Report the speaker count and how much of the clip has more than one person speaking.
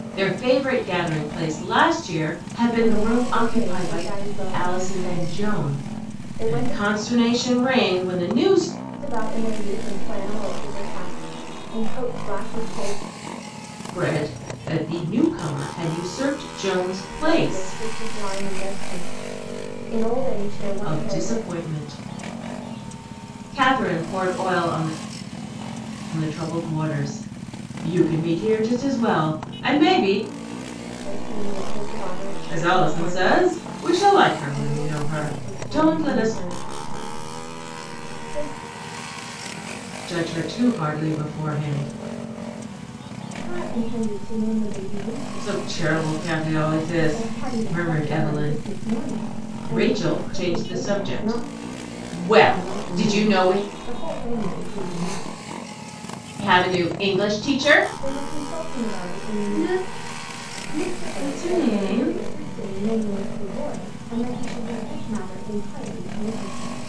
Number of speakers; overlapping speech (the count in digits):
2, about 25%